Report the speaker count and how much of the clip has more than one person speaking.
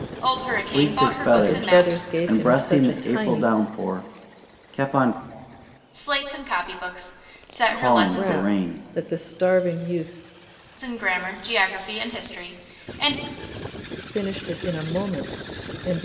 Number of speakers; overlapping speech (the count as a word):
three, about 25%